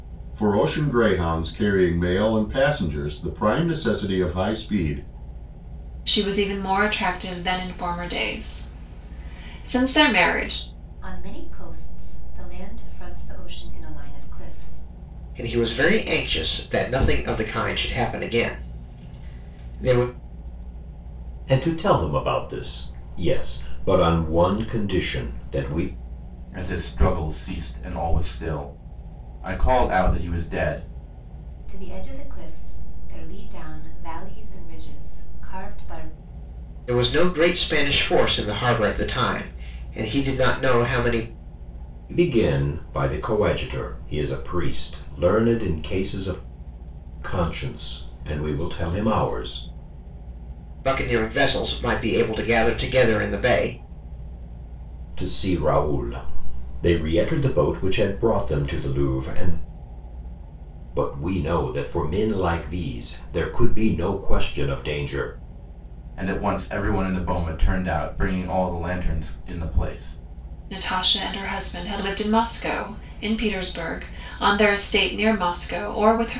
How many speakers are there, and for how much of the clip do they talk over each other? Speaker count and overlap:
6, no overlap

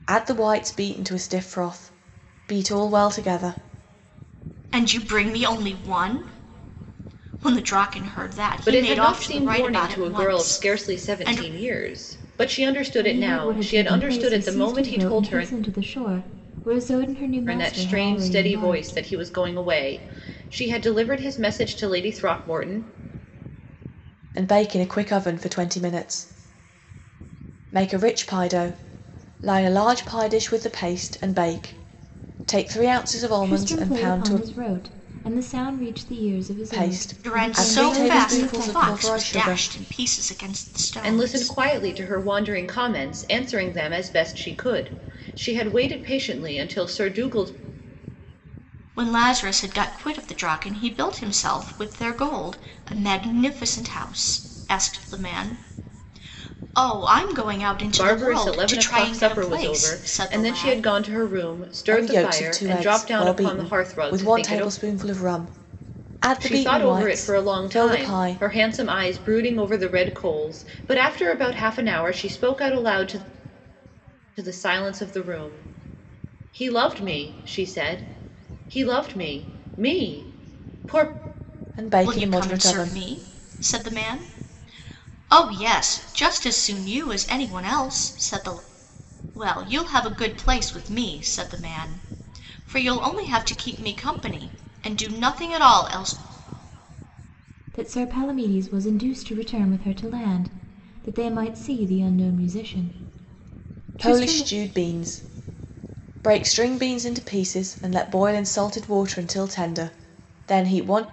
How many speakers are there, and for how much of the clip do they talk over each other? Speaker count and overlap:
4, about 19%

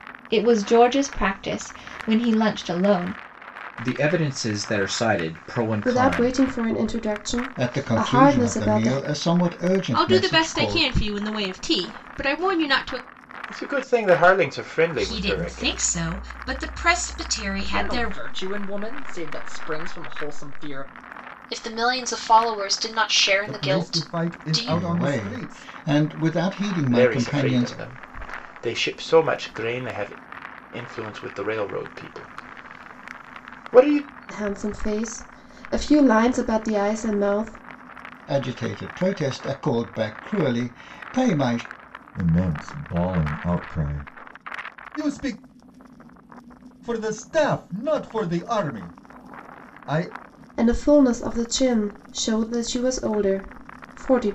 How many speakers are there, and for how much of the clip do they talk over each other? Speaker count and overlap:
10, about 14%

